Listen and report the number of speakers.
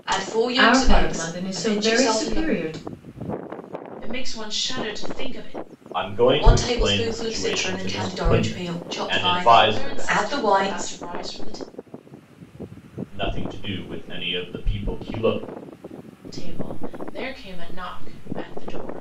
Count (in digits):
4